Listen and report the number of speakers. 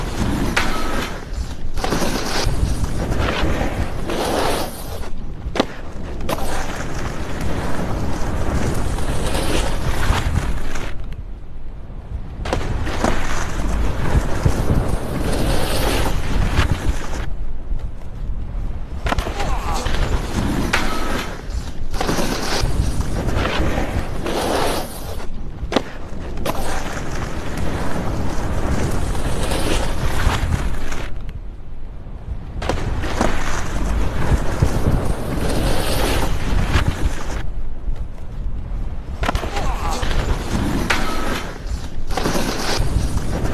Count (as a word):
zero